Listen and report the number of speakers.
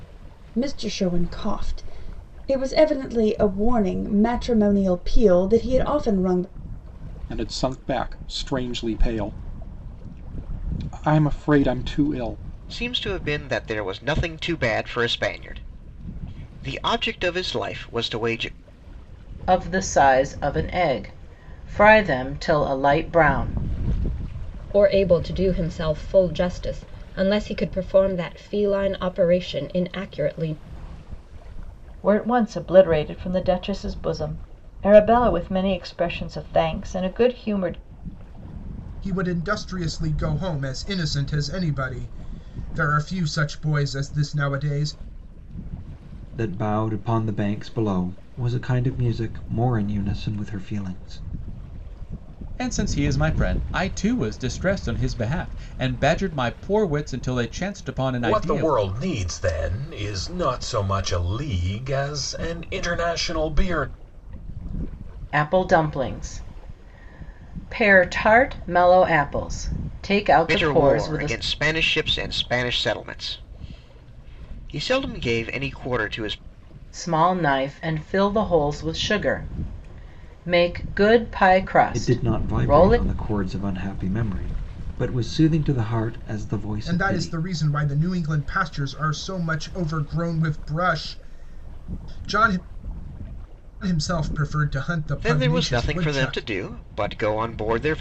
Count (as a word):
ten